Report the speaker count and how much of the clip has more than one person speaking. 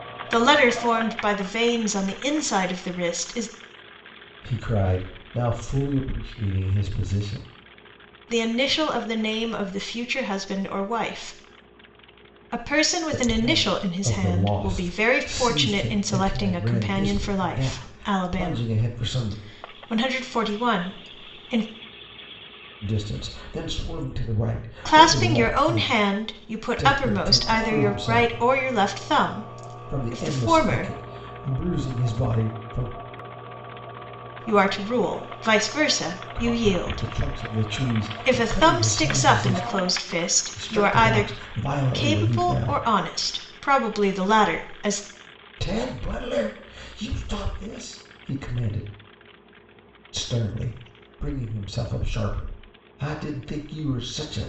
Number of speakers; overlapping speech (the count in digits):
2, about 26%